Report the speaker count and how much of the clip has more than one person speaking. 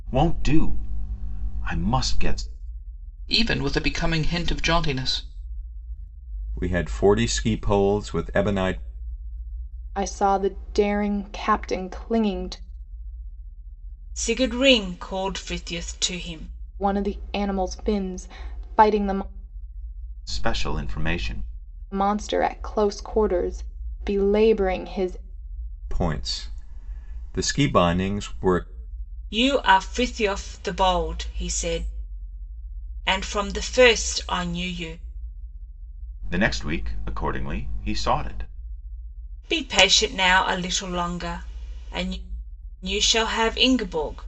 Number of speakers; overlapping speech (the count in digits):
5, no overlap